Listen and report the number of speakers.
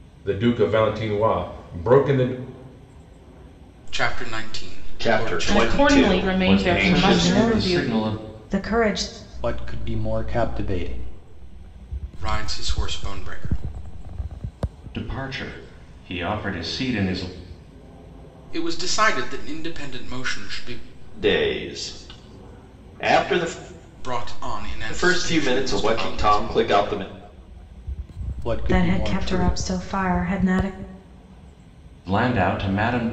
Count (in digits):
7